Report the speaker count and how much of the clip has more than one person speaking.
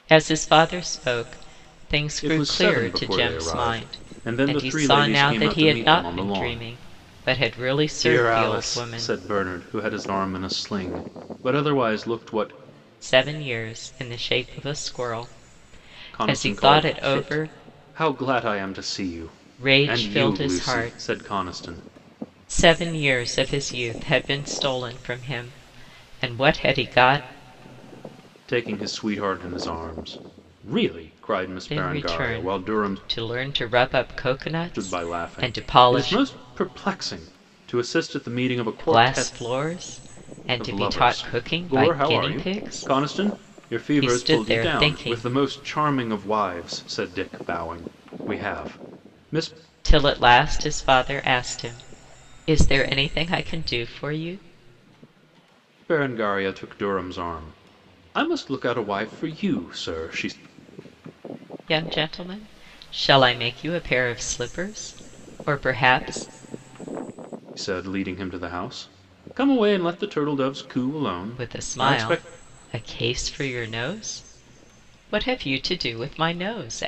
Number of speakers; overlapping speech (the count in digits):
2, about 22%